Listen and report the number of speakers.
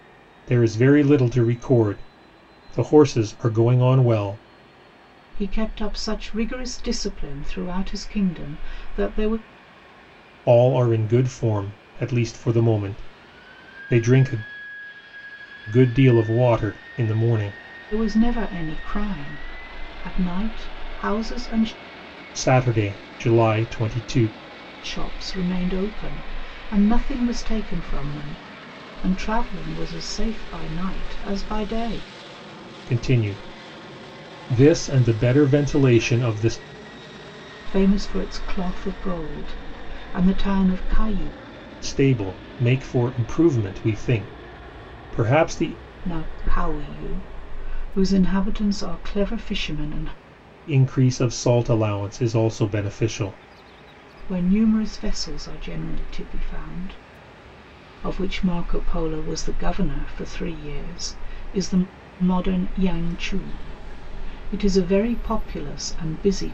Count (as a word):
two